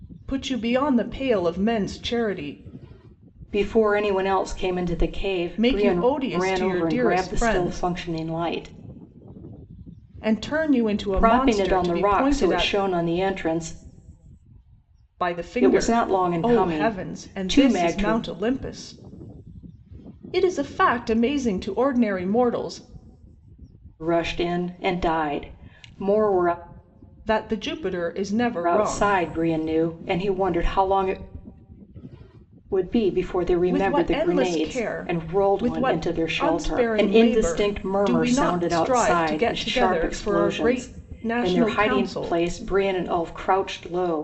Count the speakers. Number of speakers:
two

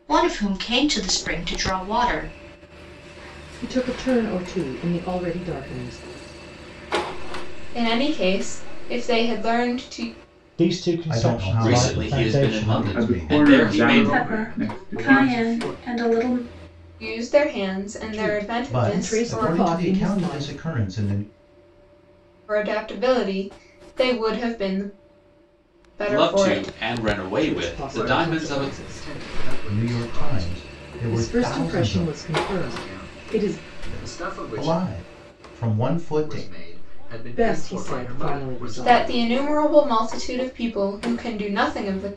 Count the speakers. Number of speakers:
ten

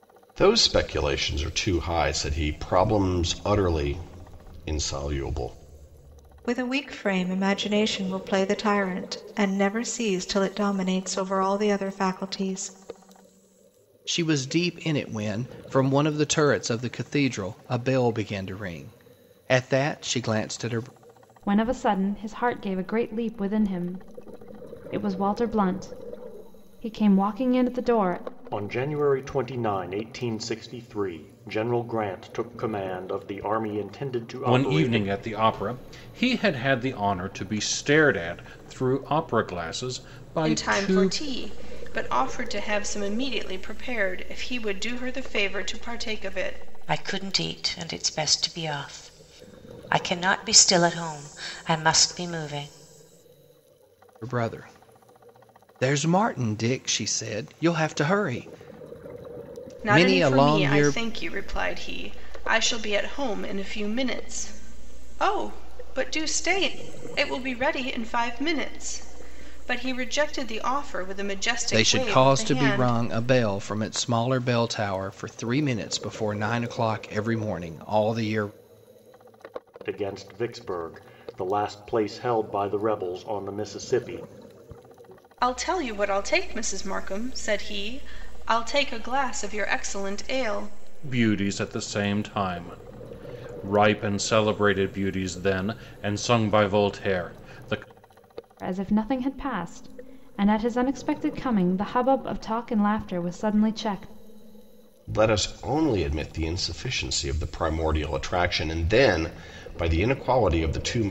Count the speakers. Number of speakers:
eight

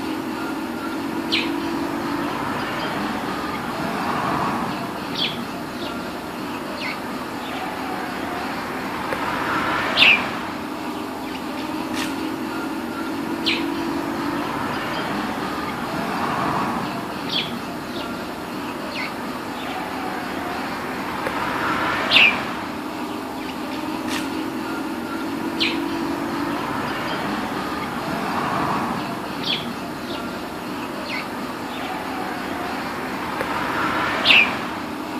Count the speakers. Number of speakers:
zero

